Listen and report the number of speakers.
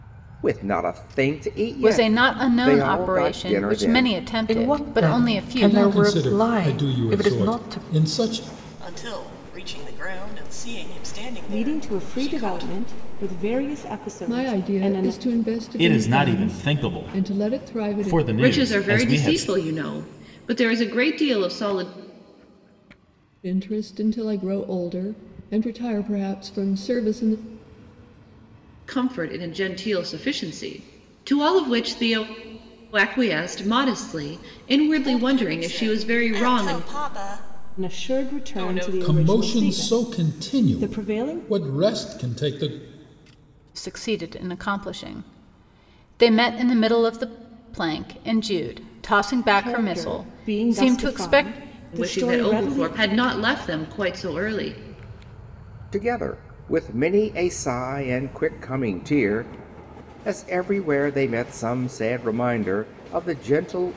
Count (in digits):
9